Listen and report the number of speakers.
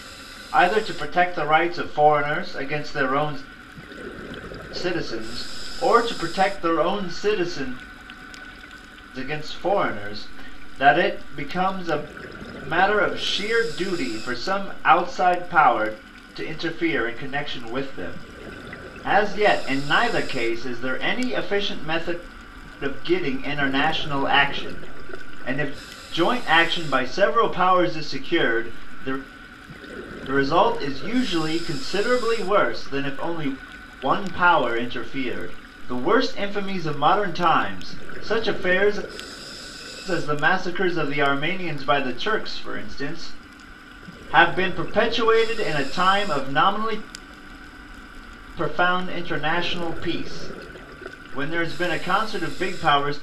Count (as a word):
one